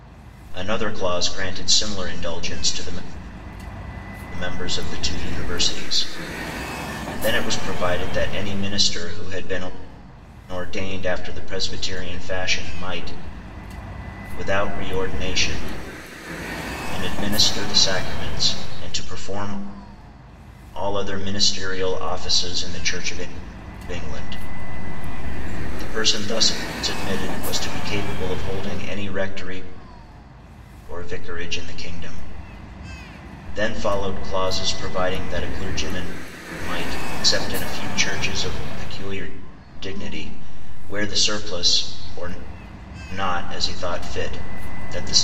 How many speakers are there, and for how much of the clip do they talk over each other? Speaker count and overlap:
1, no overlap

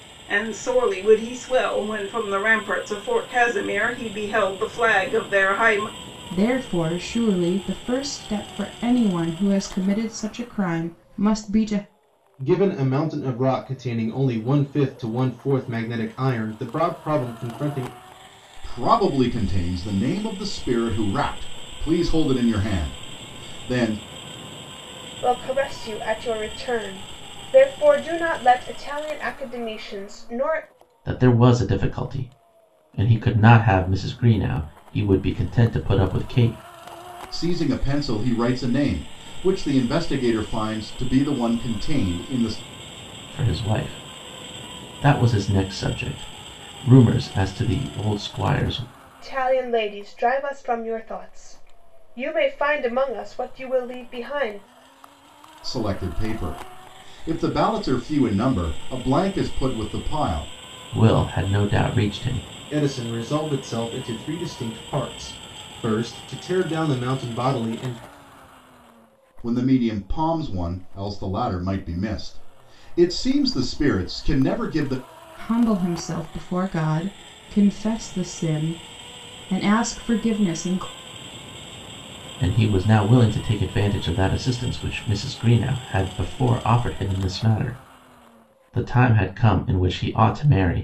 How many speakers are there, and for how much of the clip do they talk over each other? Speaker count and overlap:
6, no overlap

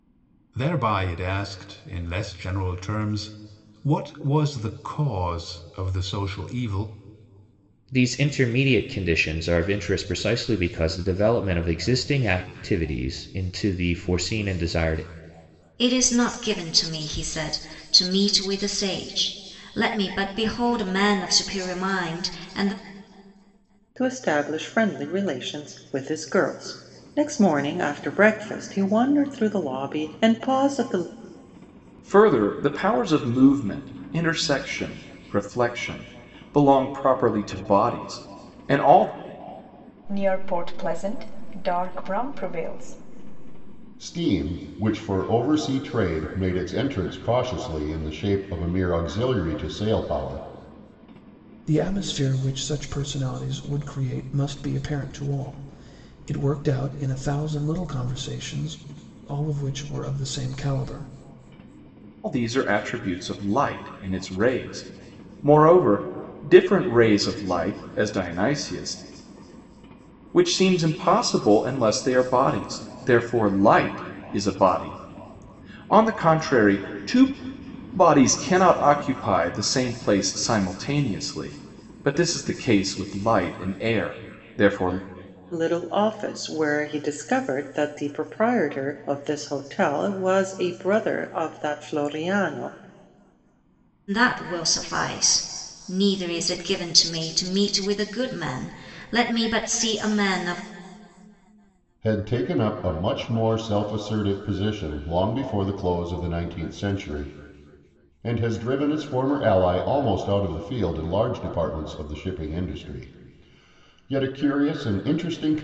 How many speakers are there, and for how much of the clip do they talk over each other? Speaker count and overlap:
8, no overlap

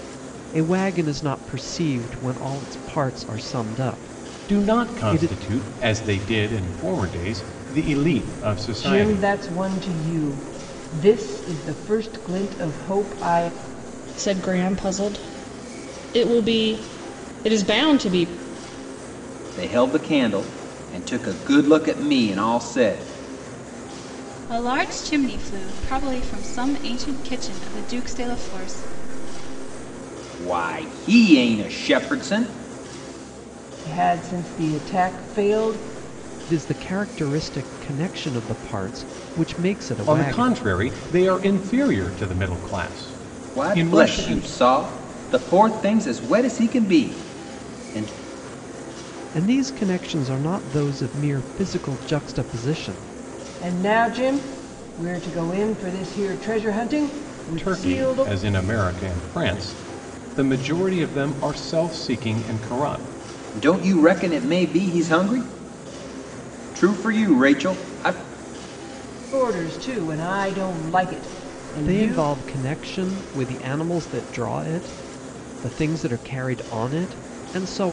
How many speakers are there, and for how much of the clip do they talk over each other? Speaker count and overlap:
6, about 5%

